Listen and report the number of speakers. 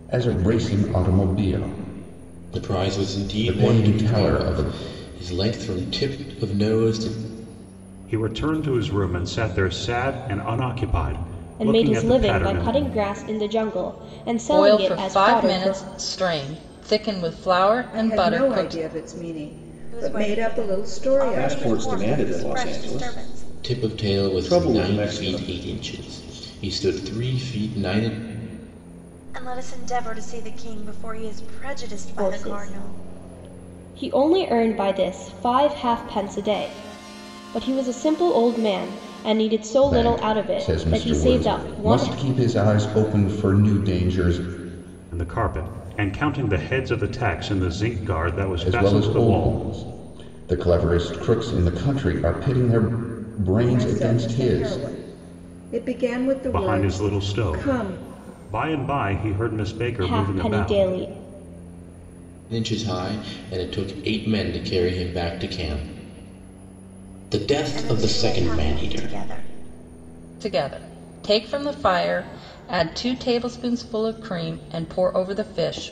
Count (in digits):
8